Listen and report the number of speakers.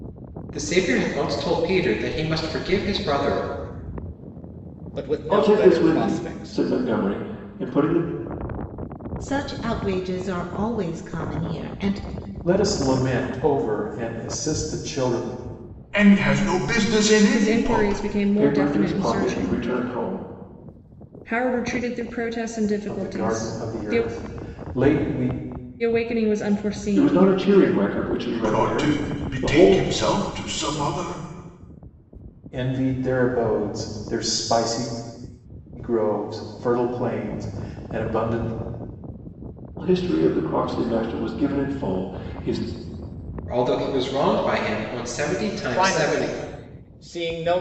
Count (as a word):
seven